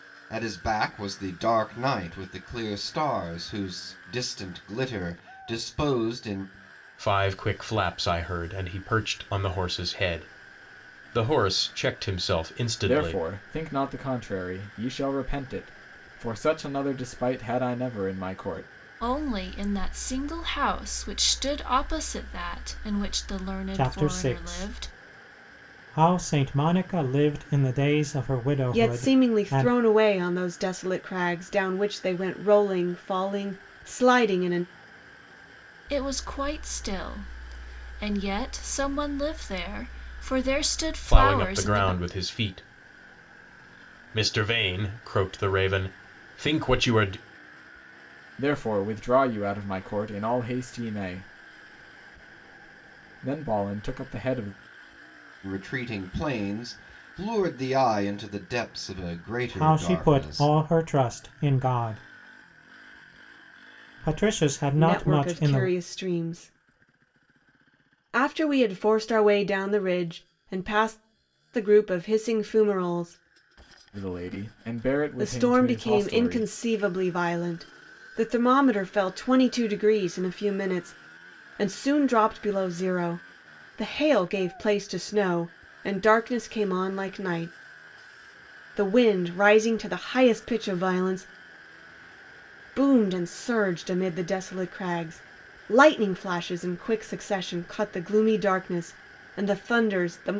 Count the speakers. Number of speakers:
6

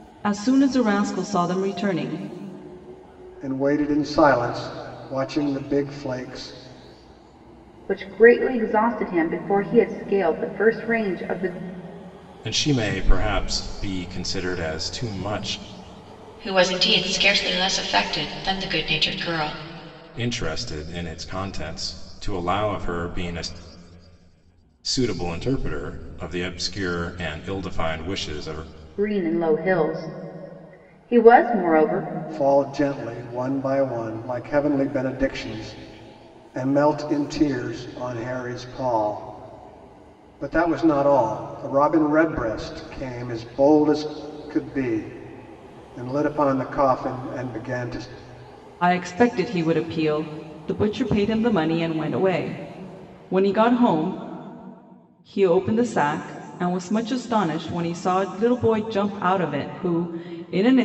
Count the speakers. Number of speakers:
5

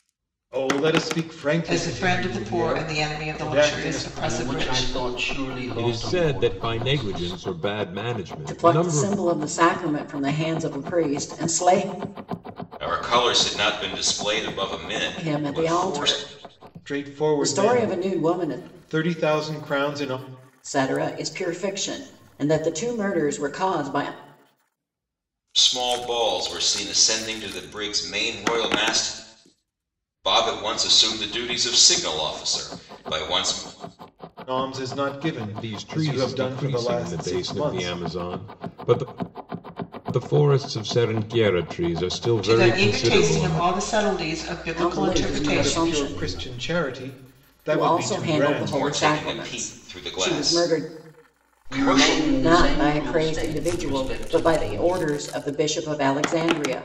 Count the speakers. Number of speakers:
6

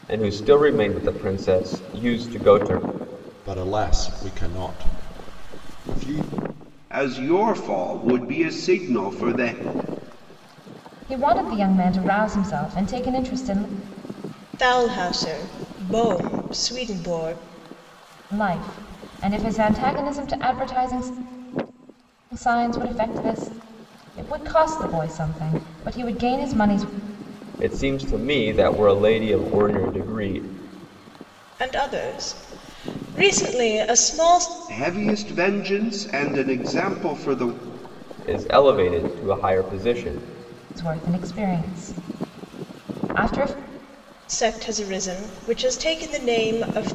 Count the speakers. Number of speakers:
5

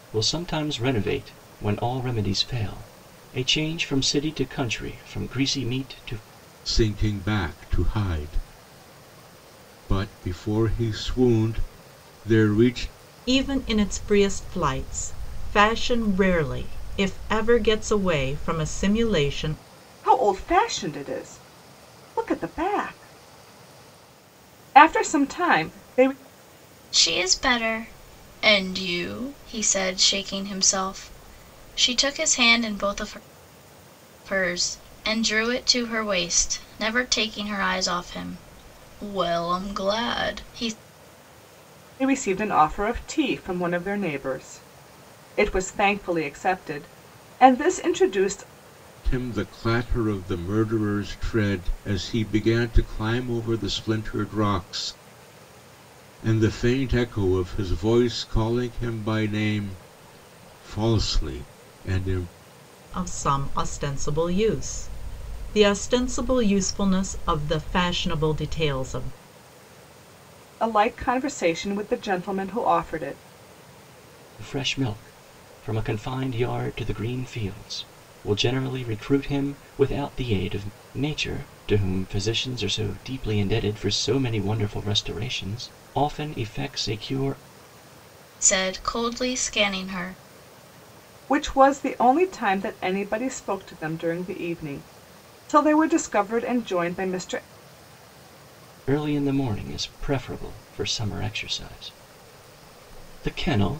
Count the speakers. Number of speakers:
5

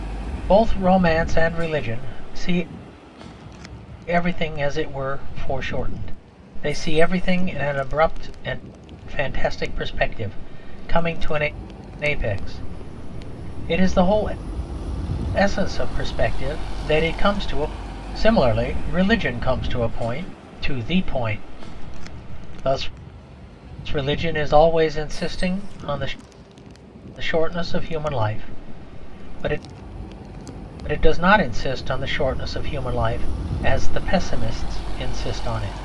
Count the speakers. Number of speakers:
1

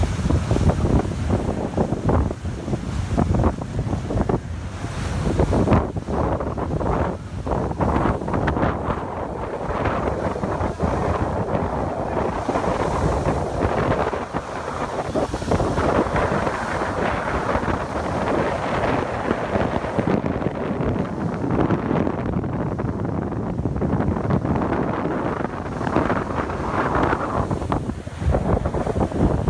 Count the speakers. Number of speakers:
0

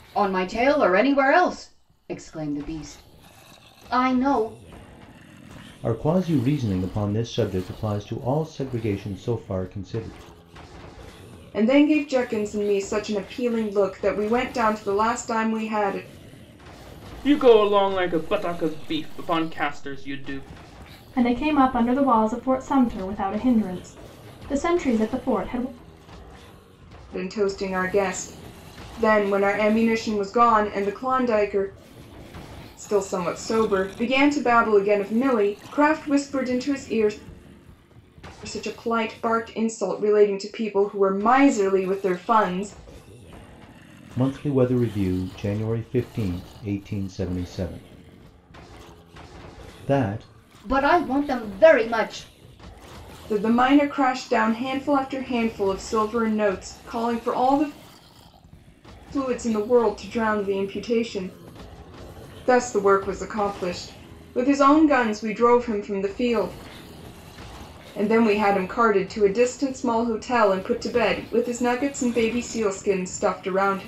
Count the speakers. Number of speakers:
5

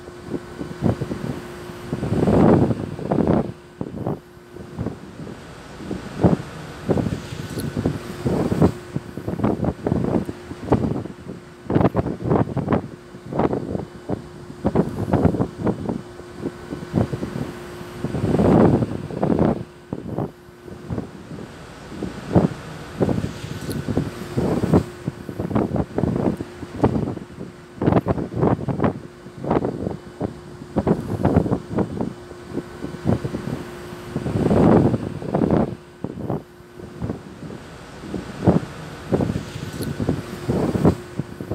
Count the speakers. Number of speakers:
0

